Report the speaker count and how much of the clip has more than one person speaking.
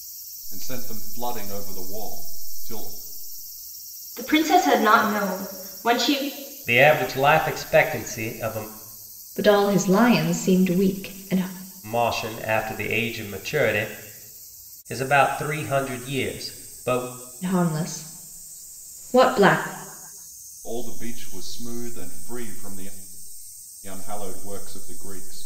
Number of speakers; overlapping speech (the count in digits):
4, no overlap